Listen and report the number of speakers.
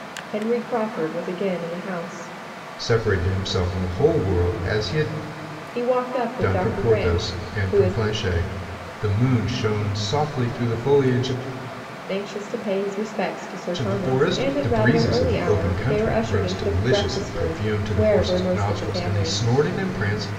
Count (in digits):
2